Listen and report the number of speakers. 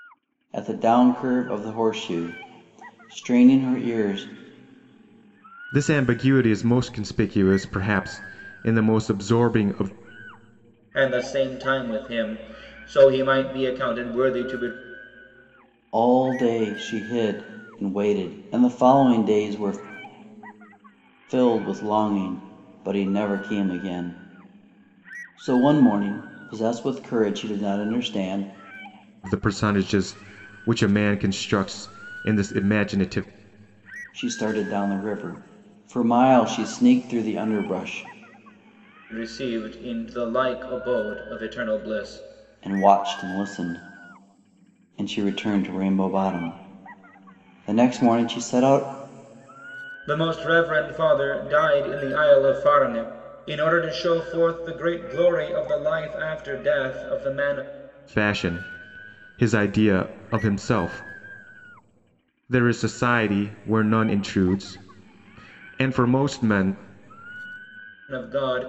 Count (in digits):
3